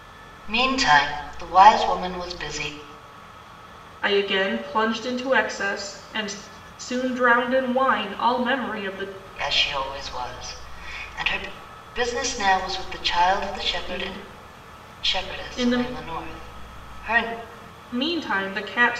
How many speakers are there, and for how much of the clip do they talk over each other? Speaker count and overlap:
two, about 7%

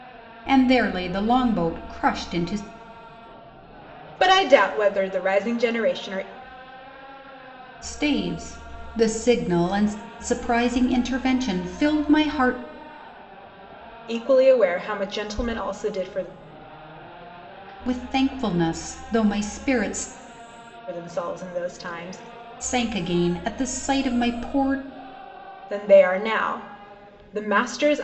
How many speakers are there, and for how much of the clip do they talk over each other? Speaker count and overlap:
two, no overlap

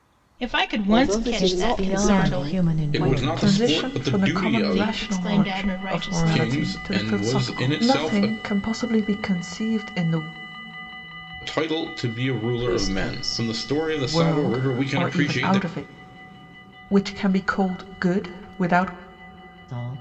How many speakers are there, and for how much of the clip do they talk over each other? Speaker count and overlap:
five, about 49%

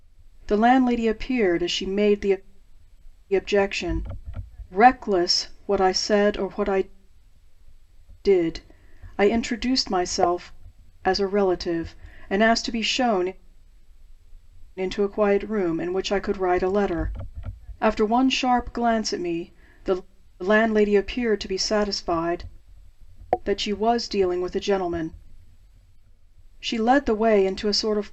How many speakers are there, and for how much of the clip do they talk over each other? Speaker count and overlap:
one, no overlap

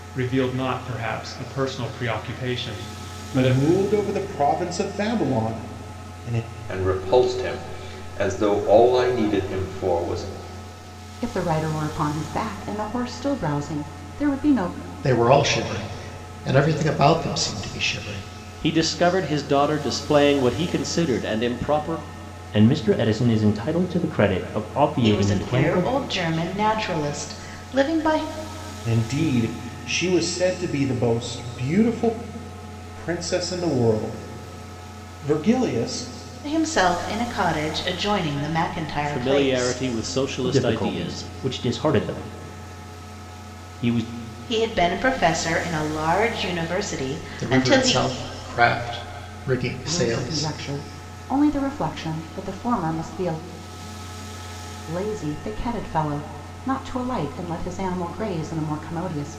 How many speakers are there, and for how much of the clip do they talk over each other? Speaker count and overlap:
eight, about 7%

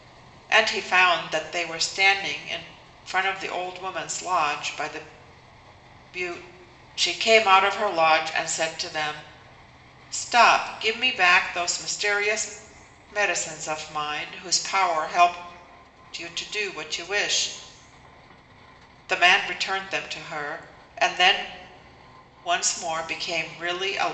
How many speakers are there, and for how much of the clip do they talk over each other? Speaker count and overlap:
one, no overlap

